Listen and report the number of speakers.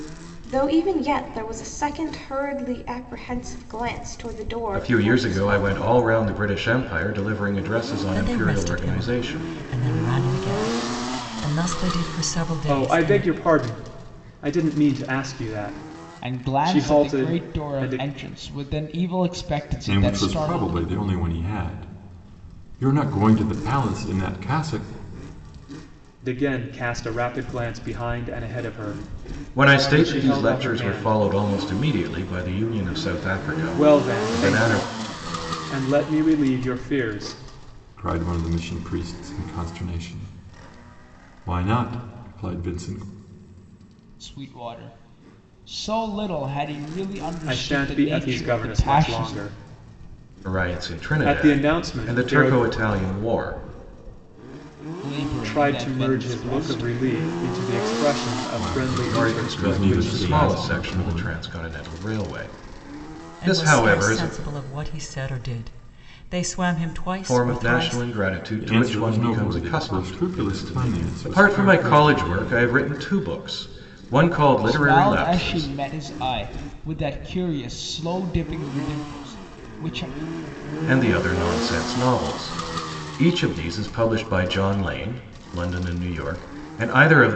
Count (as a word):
six